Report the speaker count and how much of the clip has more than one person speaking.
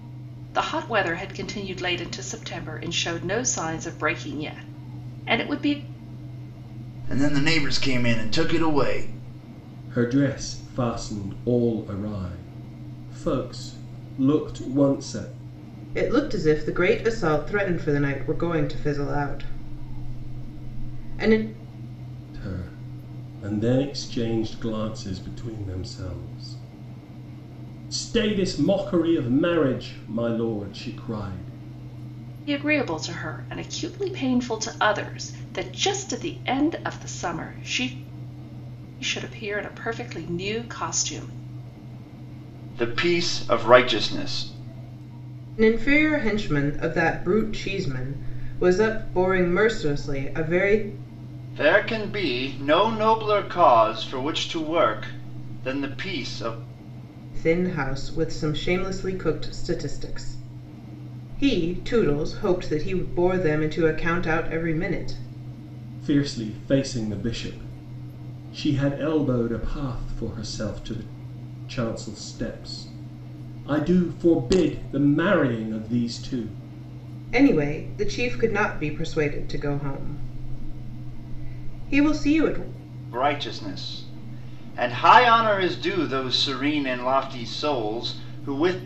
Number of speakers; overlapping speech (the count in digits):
4, no overlap